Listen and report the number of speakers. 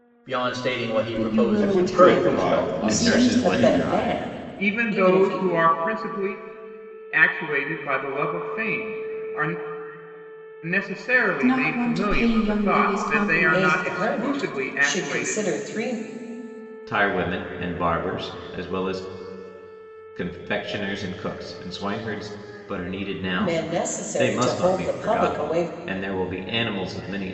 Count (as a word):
six